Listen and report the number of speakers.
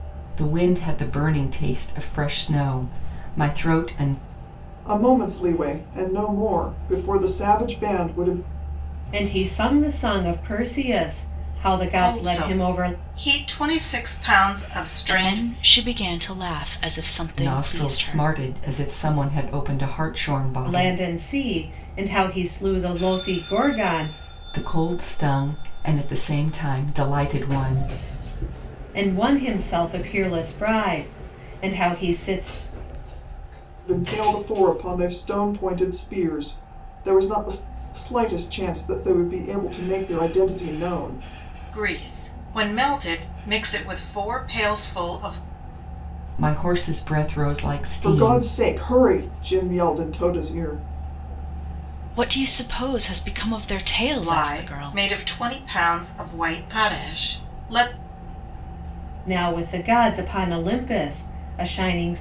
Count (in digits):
5